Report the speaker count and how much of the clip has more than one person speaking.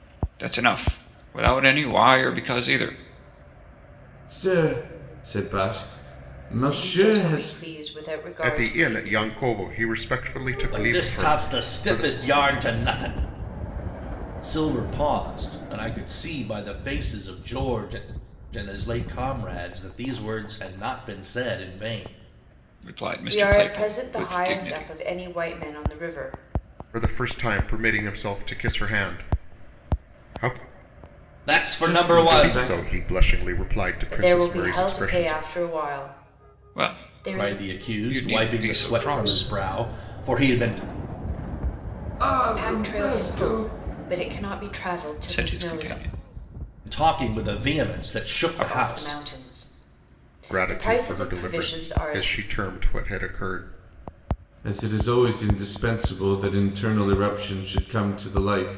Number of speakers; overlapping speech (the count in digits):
5, about 28%